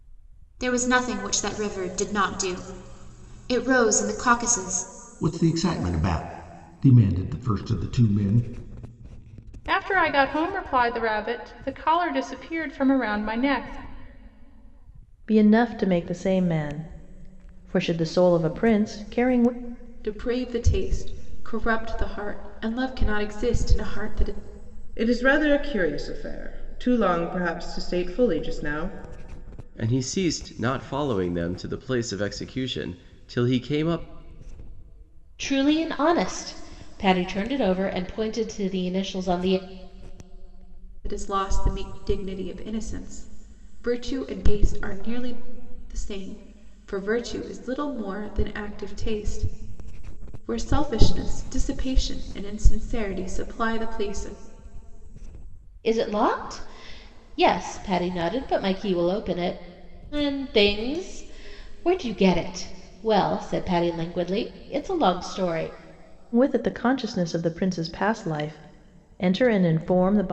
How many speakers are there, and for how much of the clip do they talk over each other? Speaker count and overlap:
eight, no overlap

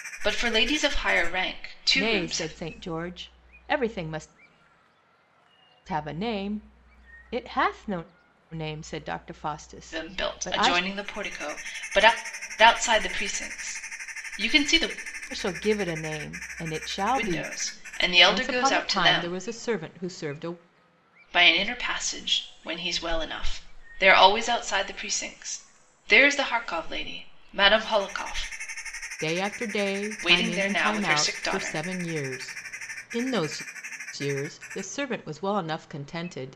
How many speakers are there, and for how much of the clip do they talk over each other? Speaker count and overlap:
two, about 13%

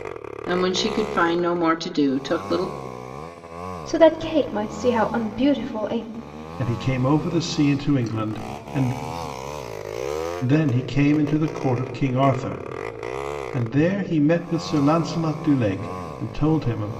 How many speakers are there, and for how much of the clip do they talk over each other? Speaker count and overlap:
three, no overlap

